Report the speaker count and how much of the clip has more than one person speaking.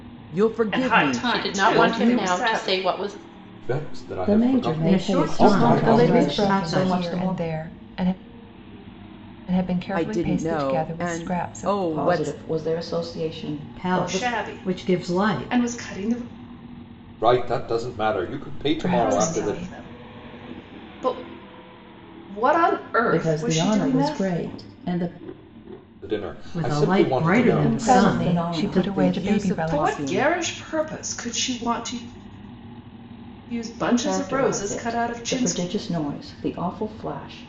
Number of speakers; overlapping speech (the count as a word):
eight, about 48%